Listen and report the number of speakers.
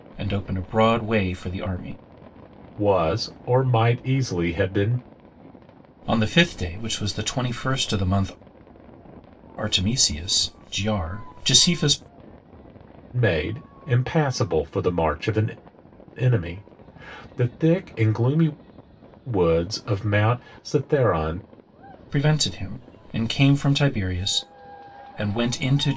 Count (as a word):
two